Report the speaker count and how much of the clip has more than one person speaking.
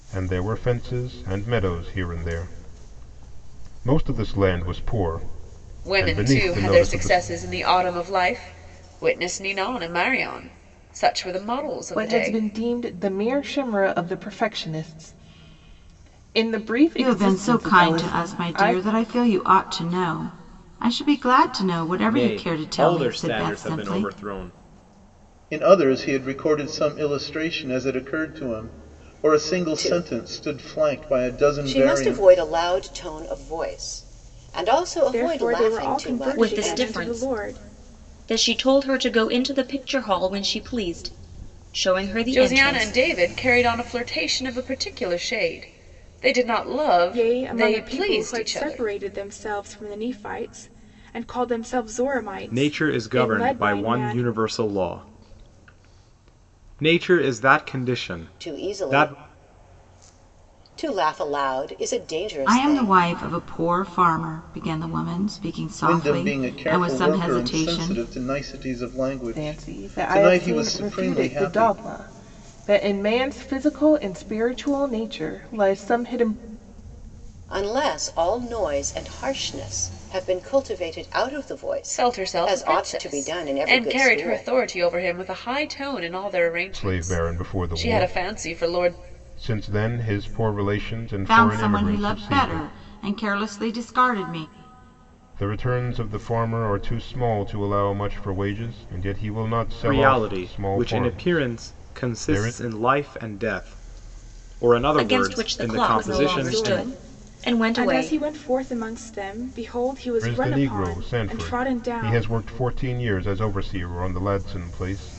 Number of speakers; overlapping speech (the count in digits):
9, about 31%